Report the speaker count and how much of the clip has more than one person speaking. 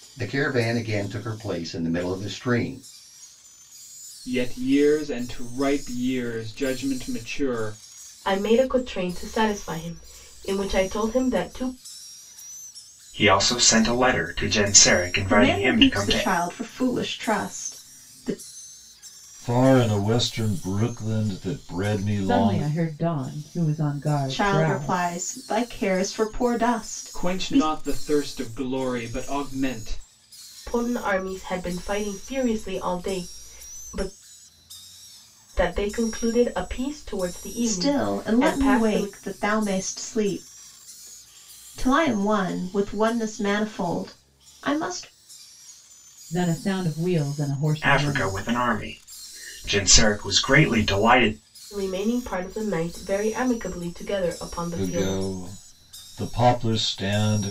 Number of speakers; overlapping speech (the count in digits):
7, about 9%